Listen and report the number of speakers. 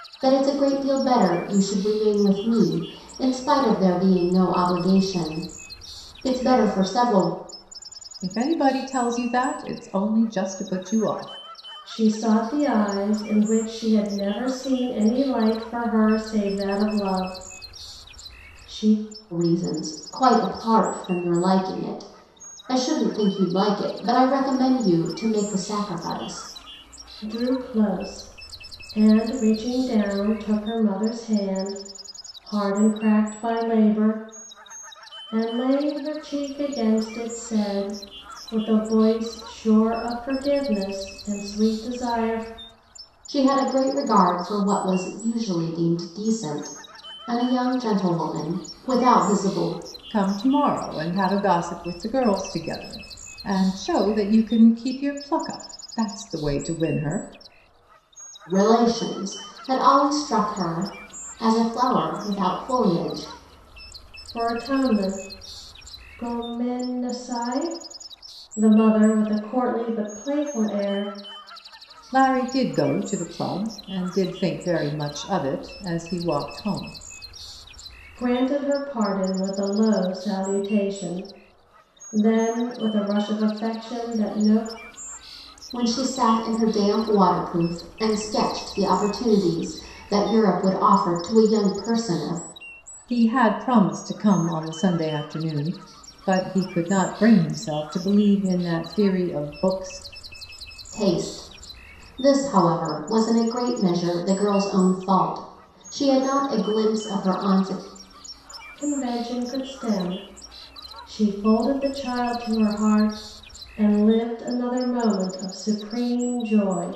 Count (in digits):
3